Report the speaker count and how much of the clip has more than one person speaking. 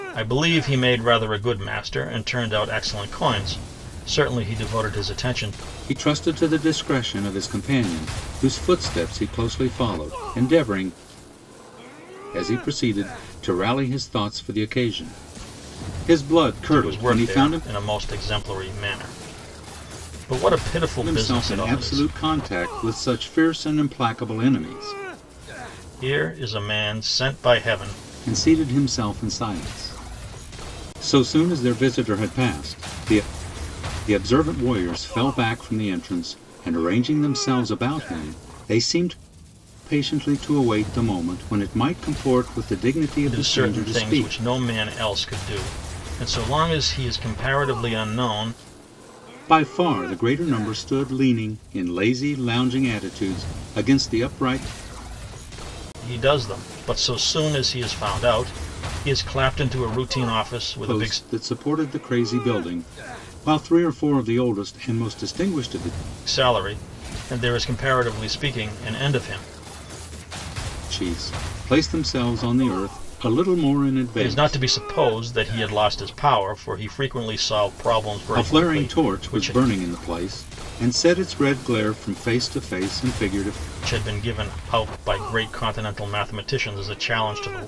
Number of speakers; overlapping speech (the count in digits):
2, about 6%